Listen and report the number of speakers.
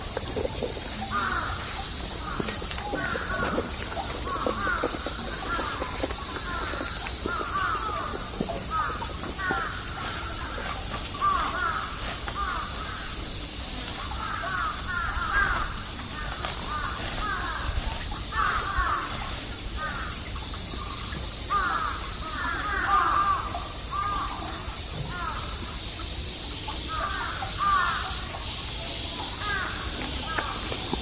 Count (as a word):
zero